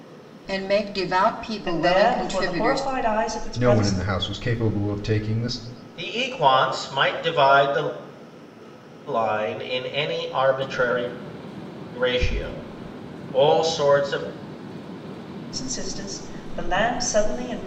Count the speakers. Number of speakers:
4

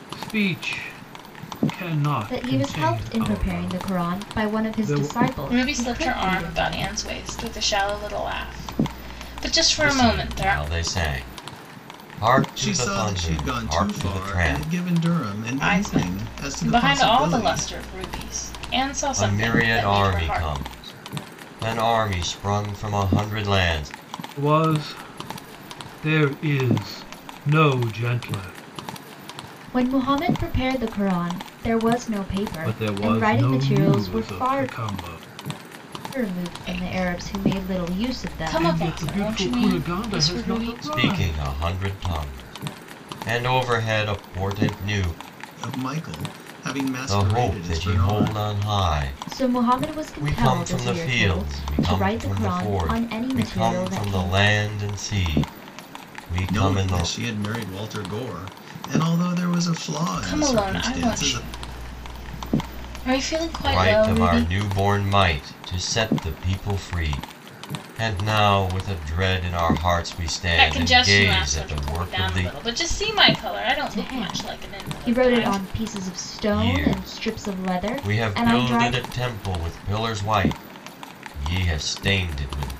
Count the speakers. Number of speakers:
5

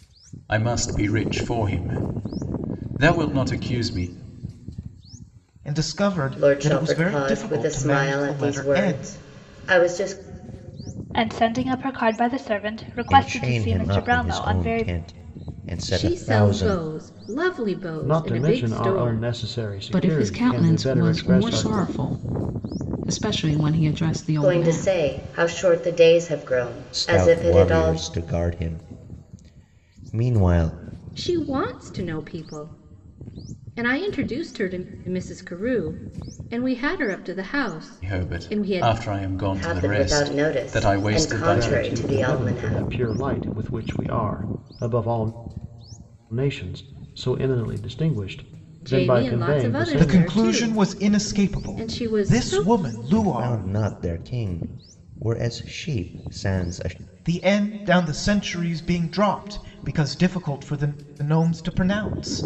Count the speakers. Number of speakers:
8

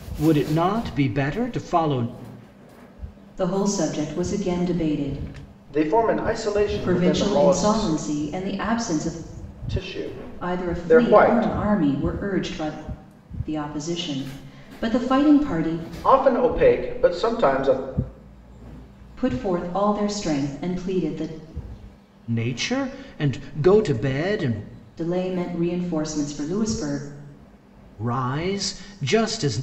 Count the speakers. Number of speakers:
3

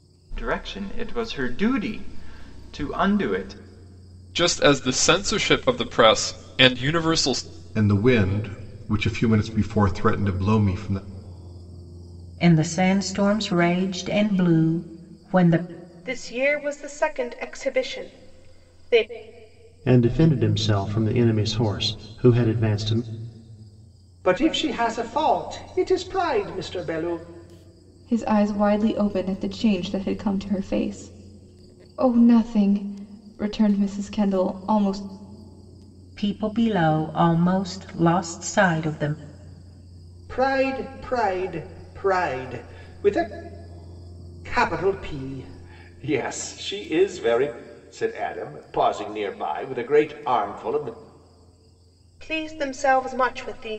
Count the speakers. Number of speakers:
8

